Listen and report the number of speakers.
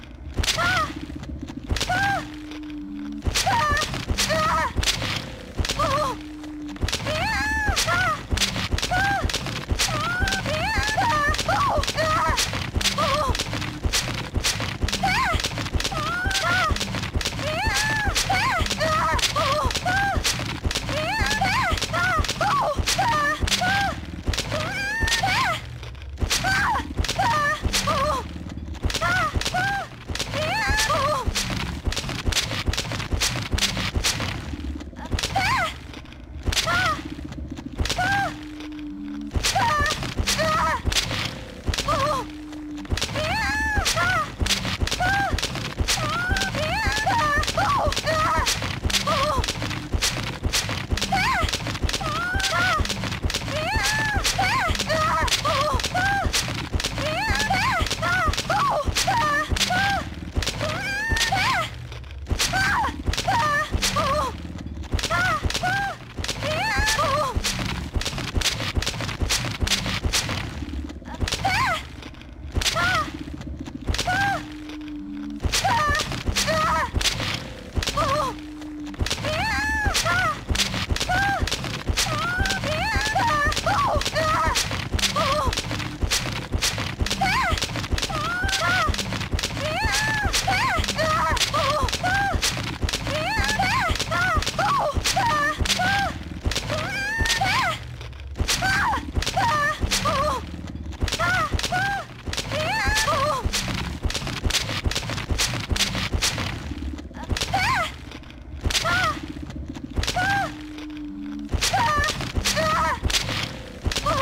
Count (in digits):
0